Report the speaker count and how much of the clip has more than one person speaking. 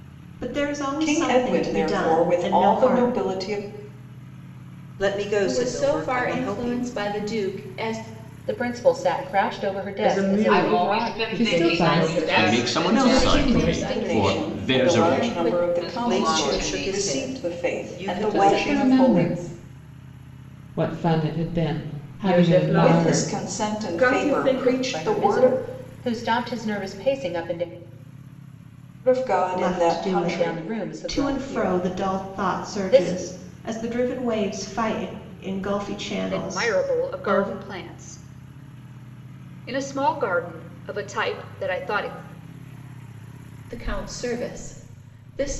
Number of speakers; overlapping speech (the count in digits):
10, about 46%